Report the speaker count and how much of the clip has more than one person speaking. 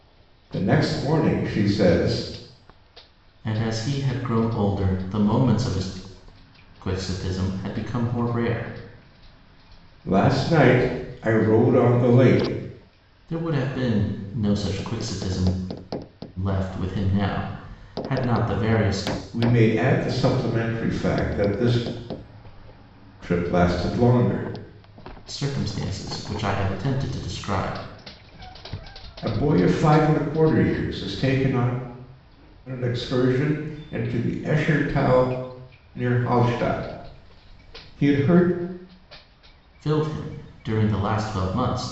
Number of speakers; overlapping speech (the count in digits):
2, no overlap